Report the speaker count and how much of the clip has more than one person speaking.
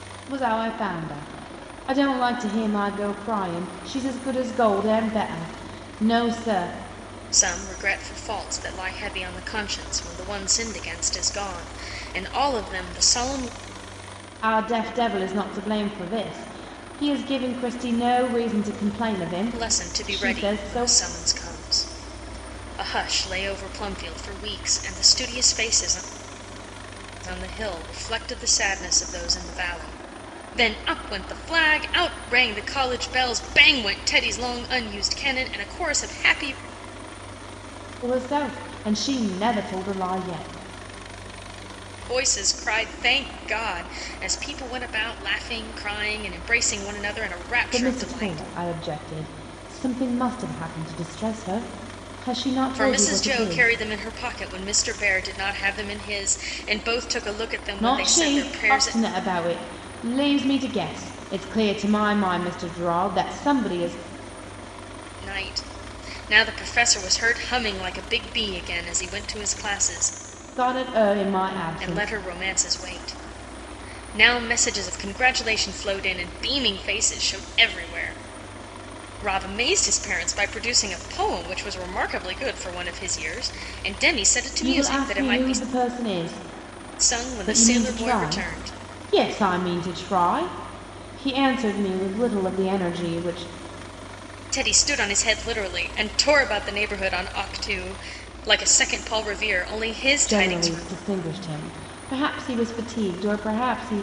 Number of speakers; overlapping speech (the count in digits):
2, about 8%